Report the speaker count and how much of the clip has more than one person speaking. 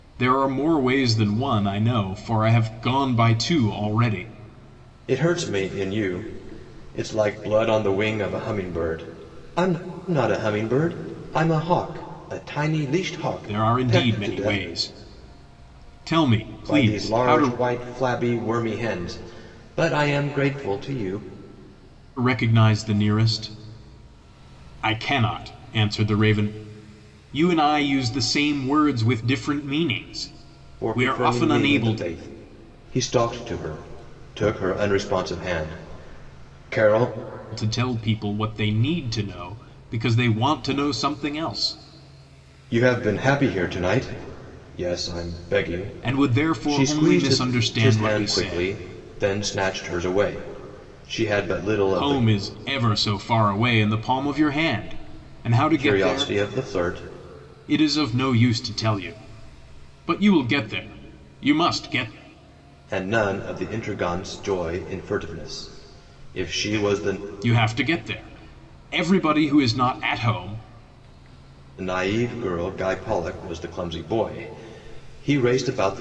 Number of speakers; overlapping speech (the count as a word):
two, about 10%